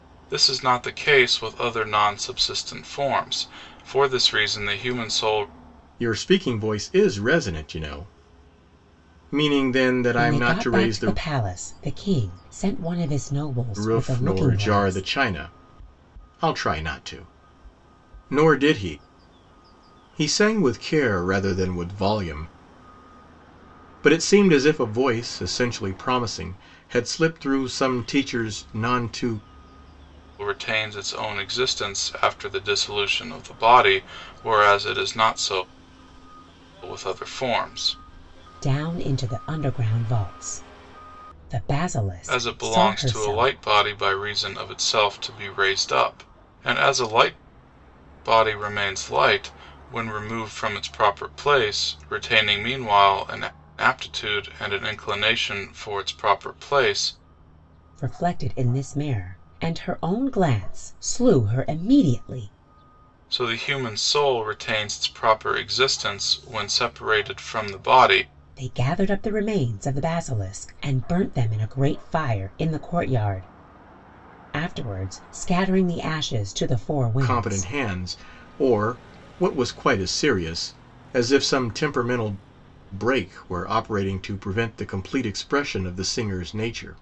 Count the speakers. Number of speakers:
3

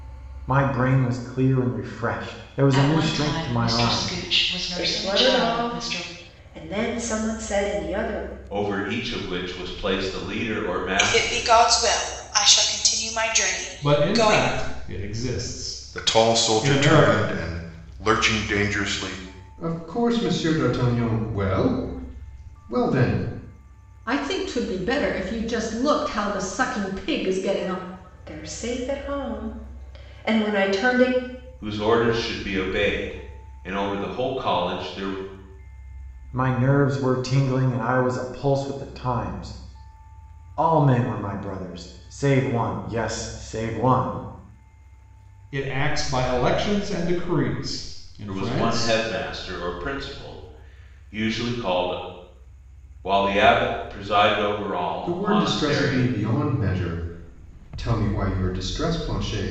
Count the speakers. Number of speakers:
9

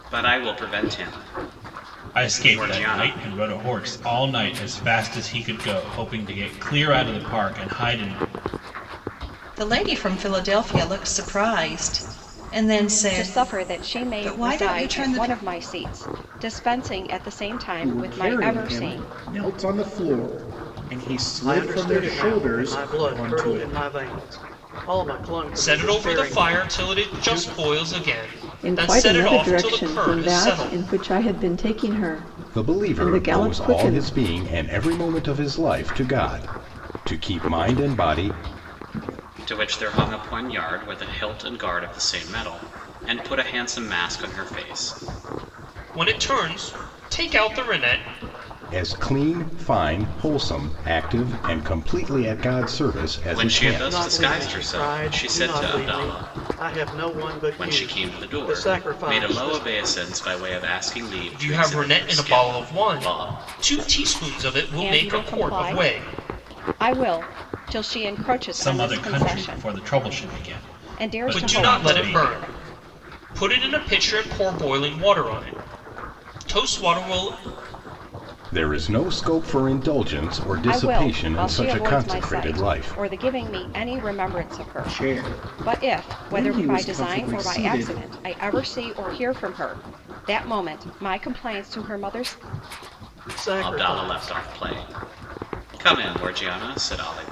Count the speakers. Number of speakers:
9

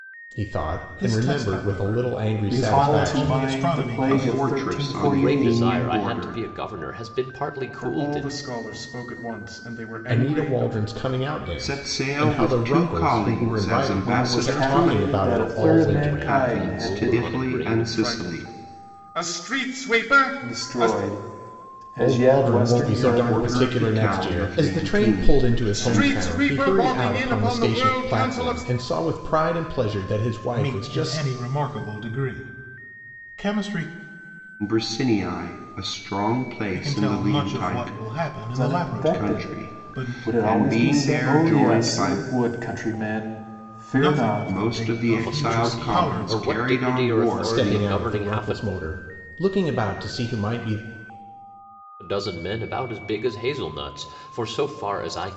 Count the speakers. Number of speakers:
6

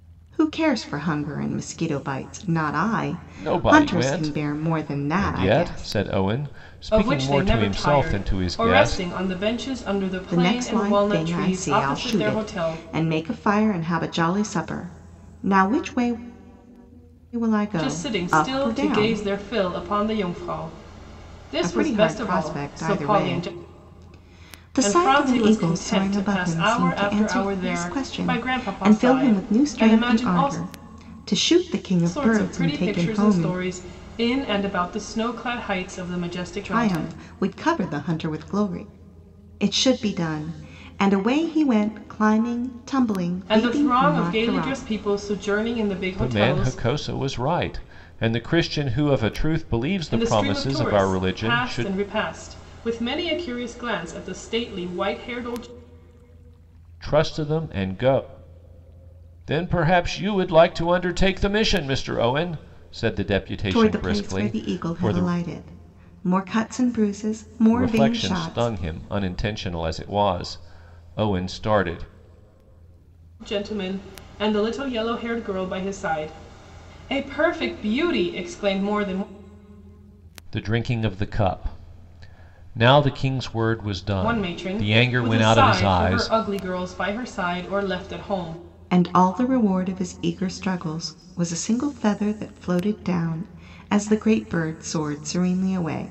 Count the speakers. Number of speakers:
3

